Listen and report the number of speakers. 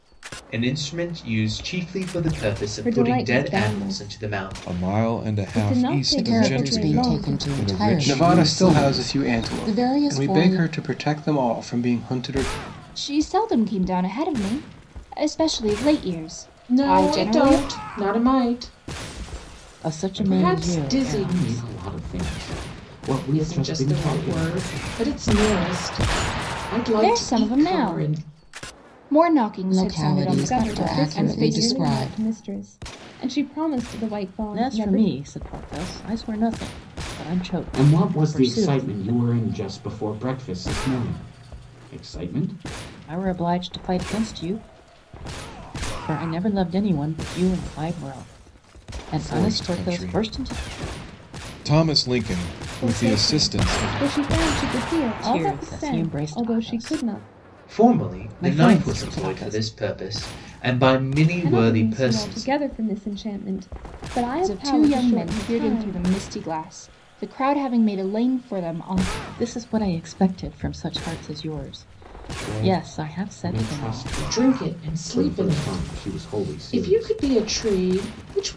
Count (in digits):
9